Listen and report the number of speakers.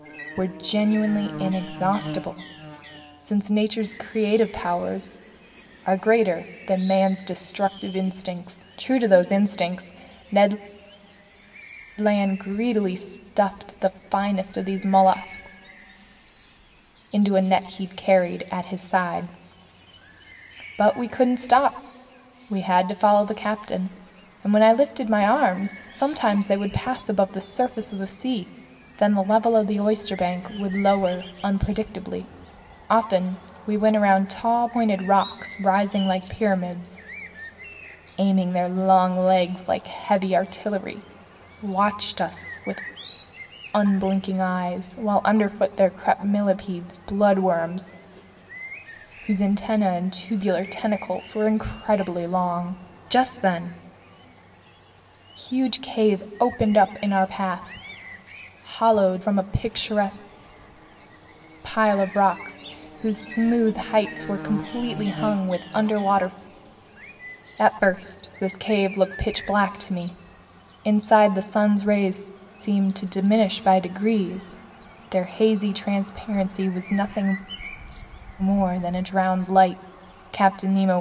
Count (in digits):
1